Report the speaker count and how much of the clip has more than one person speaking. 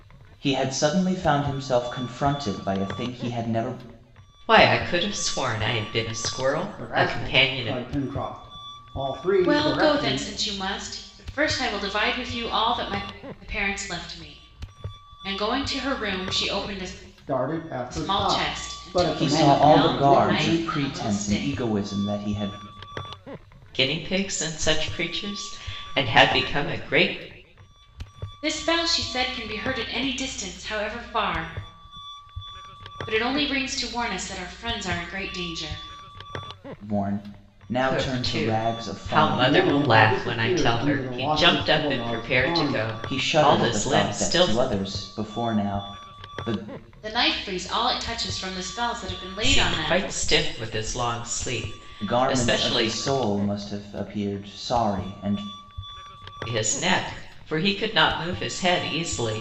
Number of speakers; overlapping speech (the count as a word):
four, about 23%